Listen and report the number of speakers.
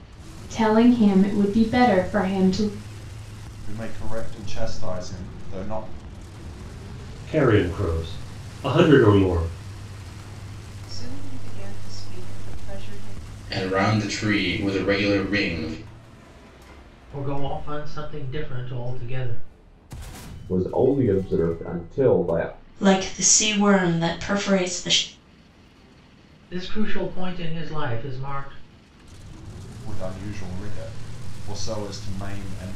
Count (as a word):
eight